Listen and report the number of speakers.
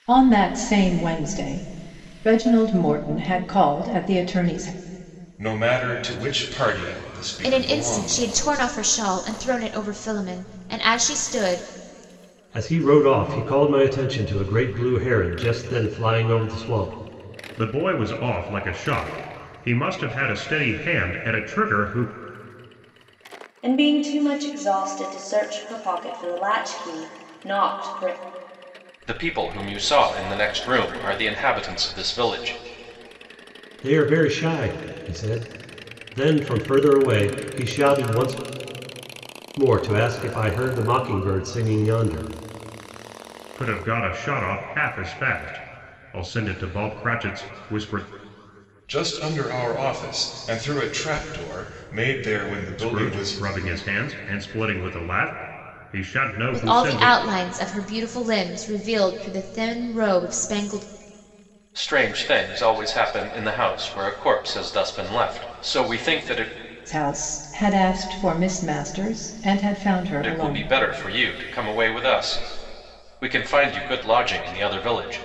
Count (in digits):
7